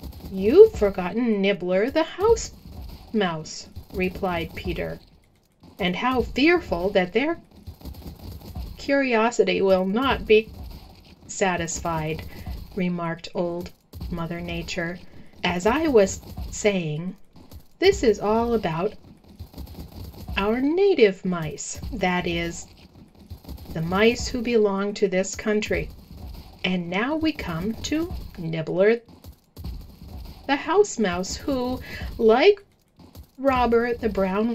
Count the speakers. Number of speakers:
one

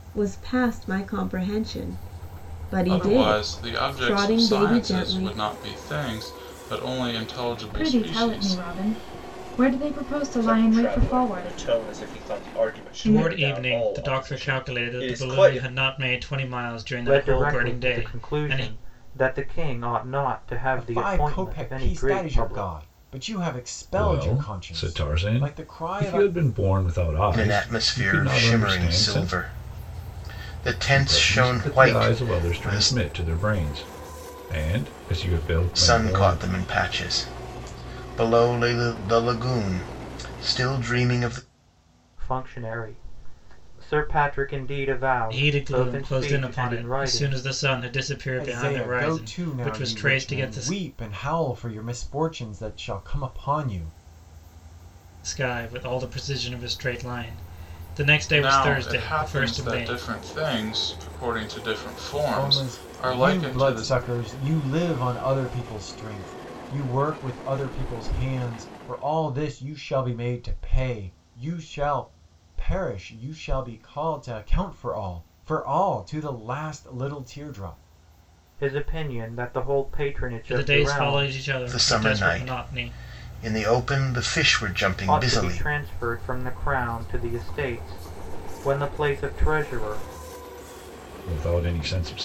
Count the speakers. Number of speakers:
nine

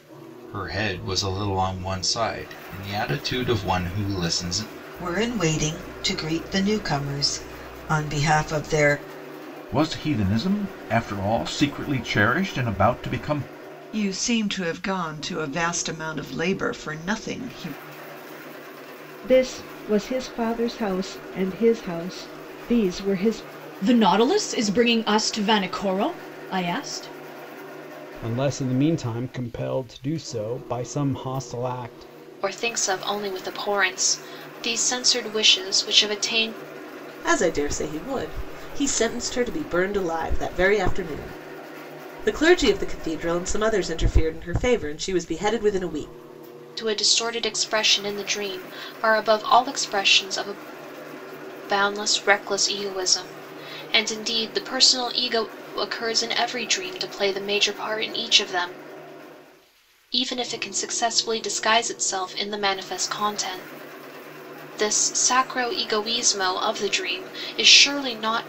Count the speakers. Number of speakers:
nine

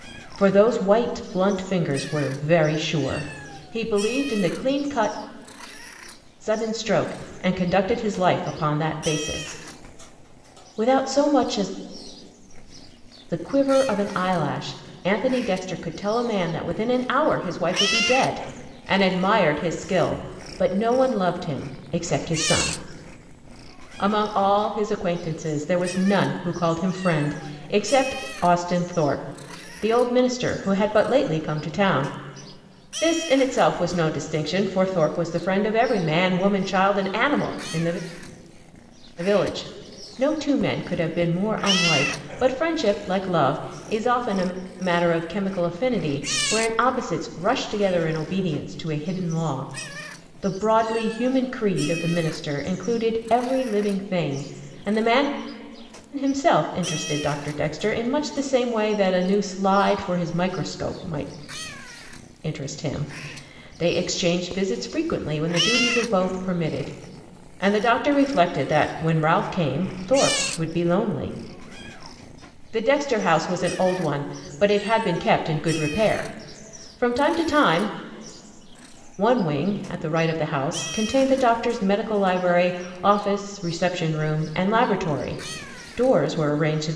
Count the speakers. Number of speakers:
one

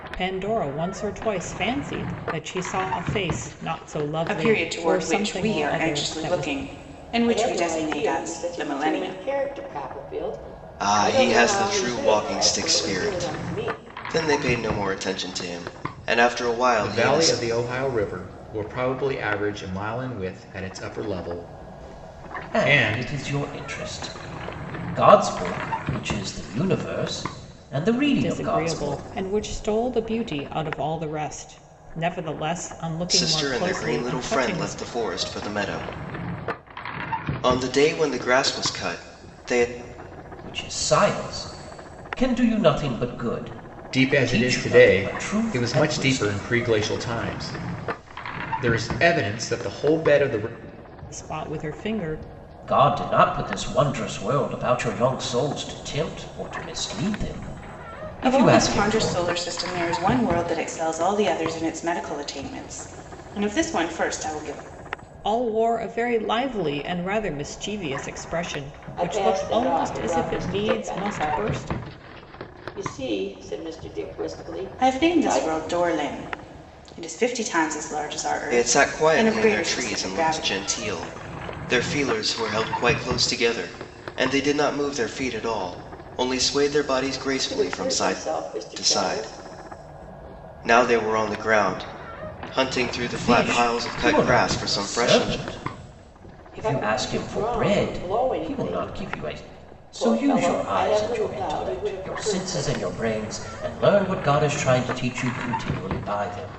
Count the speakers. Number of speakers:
six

